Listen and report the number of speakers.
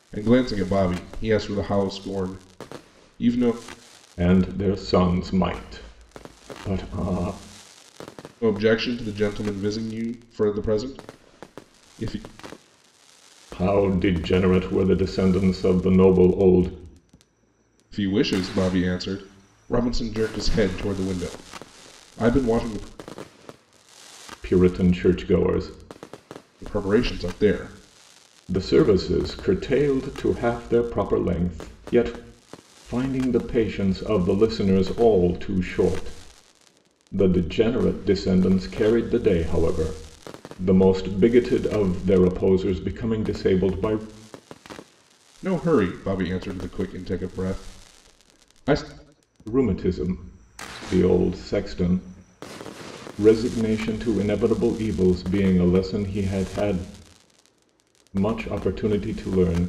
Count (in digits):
2